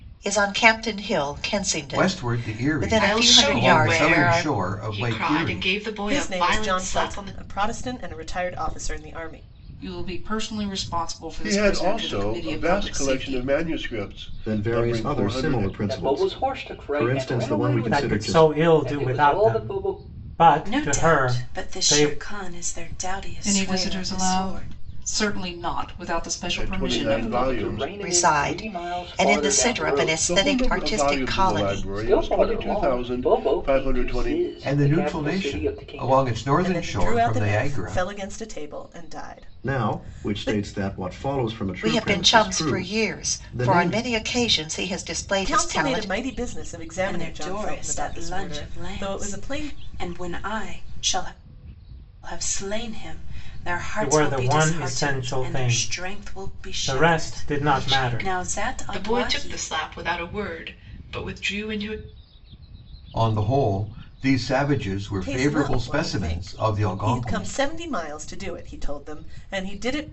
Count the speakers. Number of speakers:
10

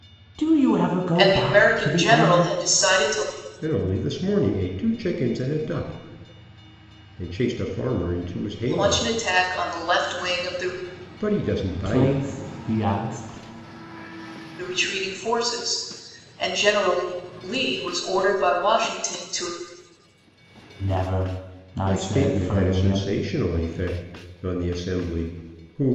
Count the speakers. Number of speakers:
3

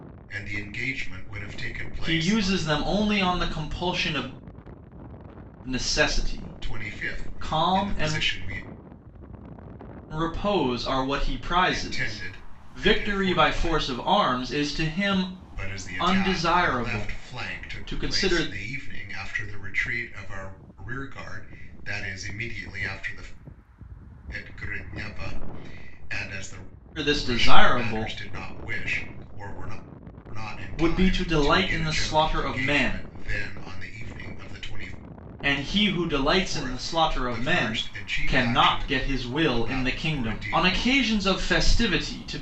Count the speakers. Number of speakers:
2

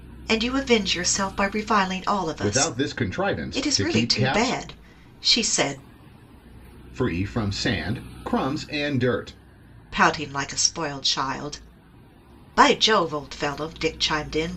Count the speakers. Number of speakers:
2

